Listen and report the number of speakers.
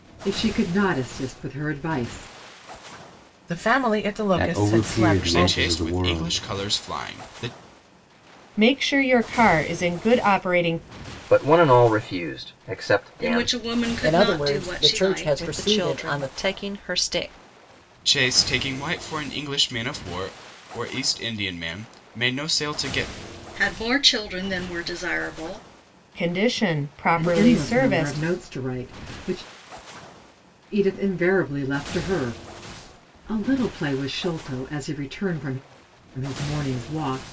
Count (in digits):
9